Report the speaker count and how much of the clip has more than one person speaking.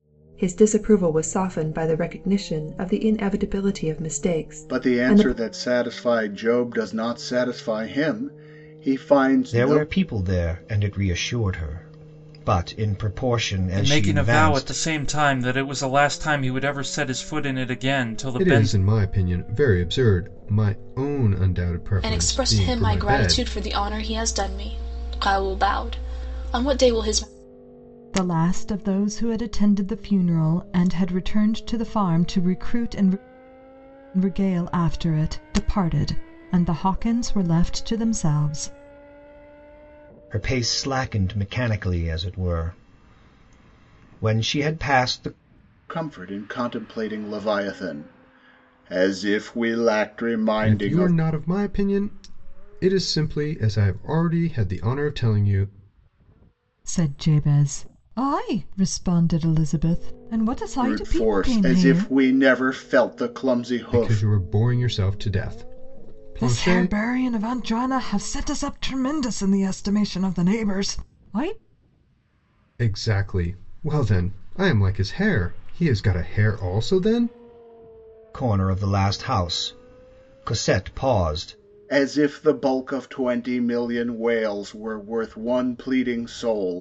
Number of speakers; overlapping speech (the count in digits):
7, about 8%